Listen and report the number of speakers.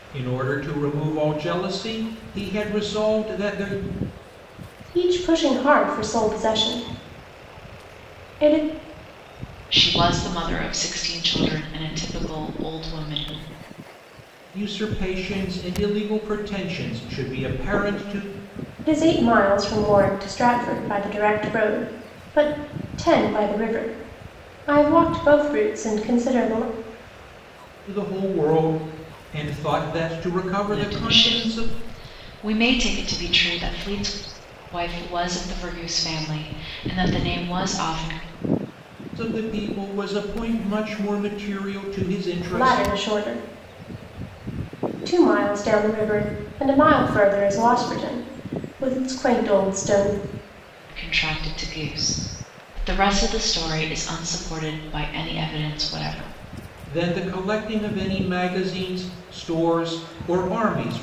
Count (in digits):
3